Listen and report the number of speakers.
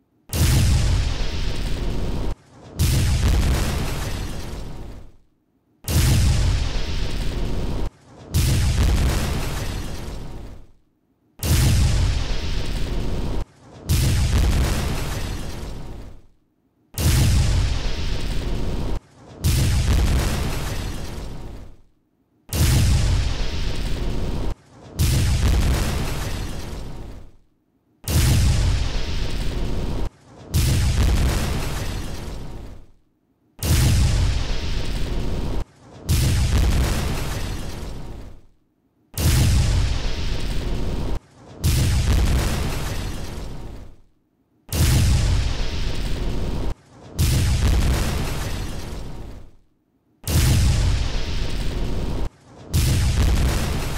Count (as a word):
zero